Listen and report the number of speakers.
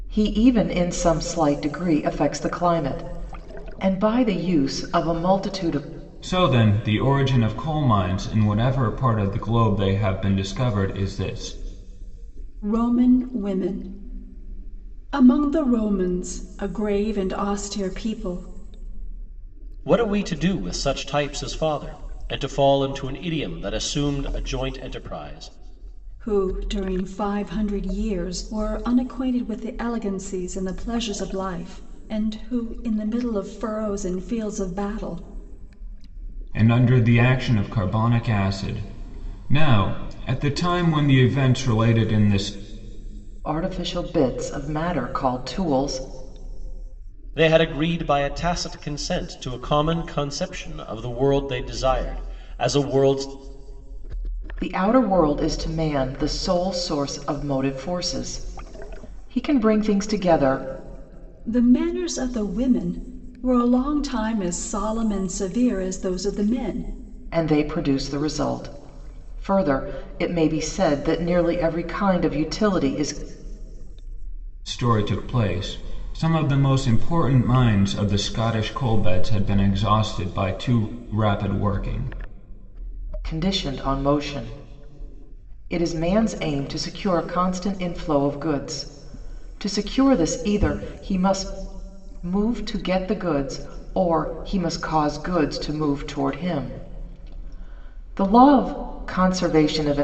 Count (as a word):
four